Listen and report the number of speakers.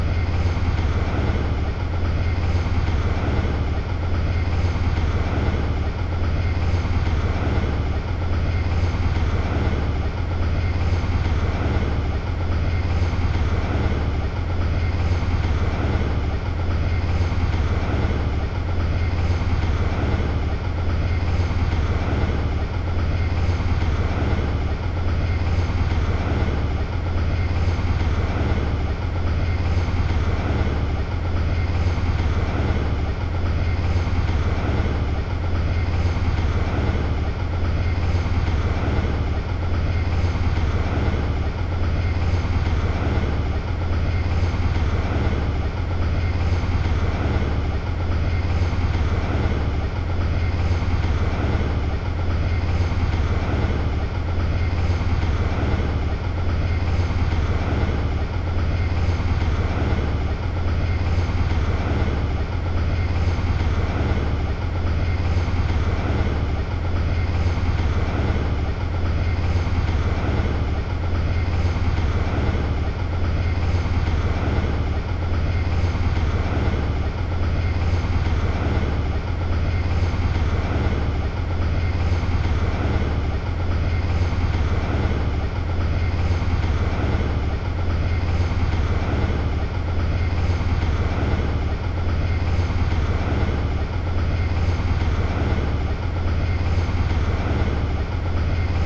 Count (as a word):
zero